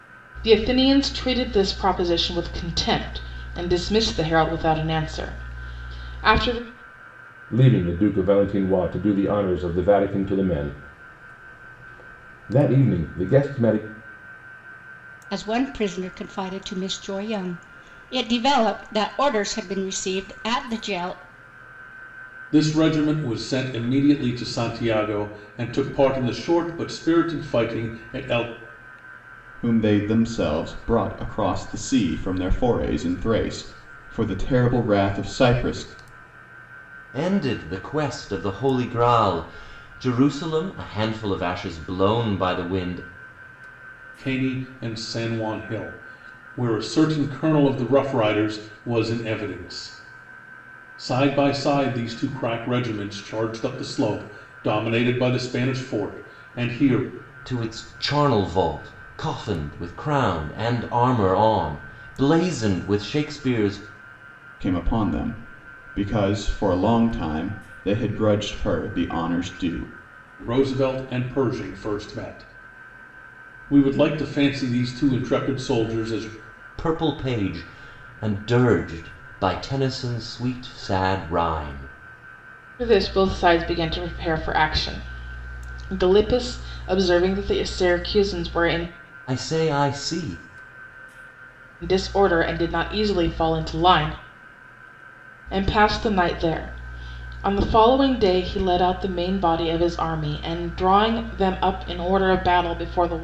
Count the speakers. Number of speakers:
six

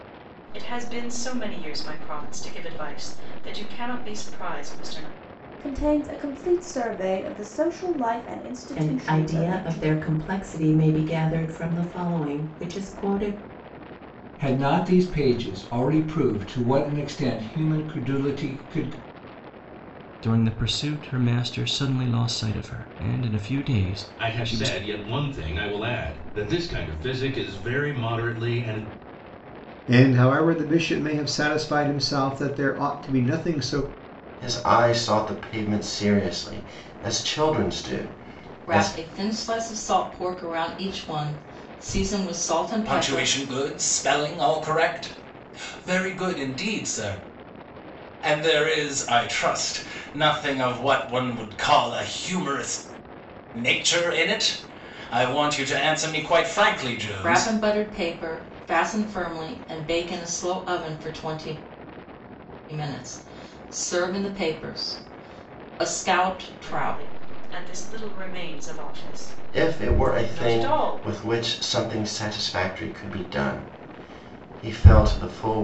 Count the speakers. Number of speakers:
ten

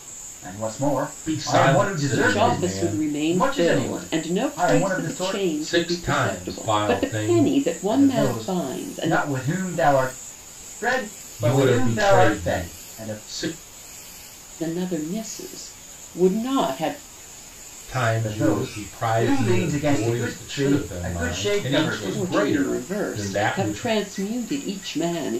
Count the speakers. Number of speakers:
three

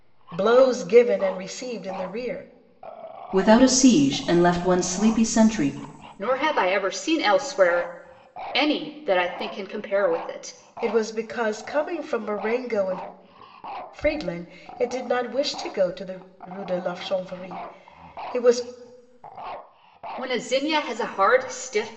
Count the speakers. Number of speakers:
three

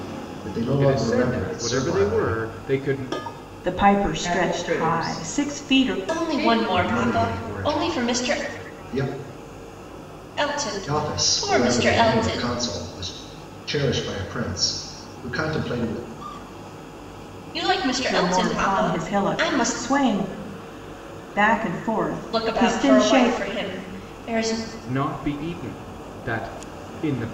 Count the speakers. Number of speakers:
five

